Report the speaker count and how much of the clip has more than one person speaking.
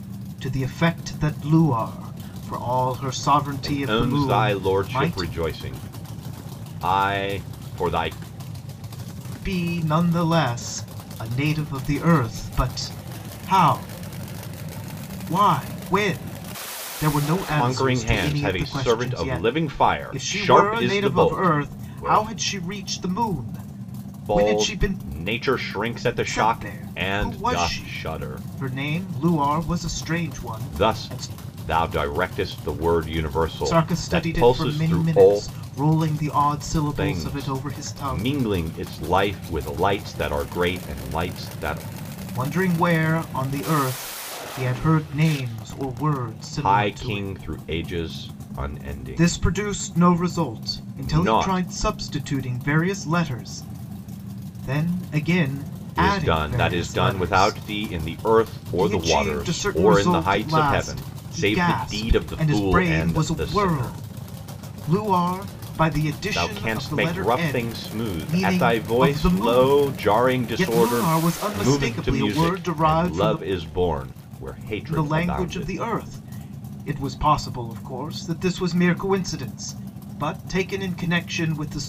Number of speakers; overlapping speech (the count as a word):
two, about 37%